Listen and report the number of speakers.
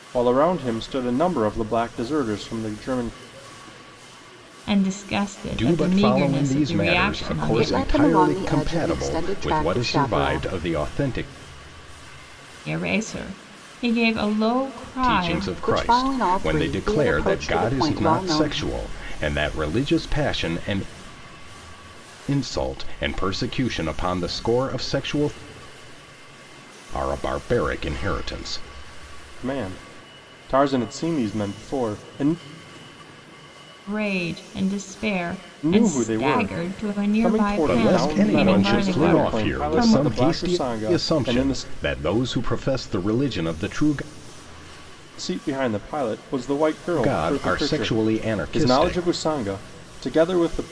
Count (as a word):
four